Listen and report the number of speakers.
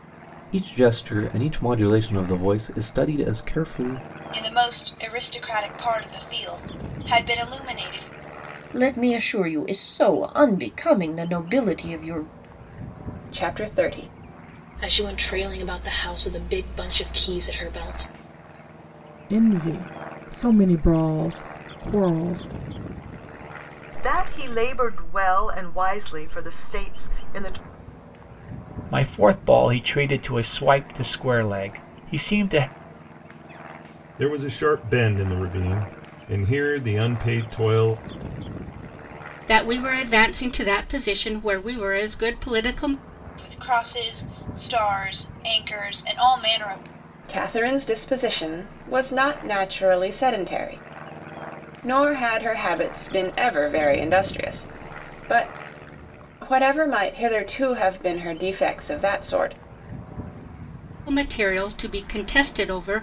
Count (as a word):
ten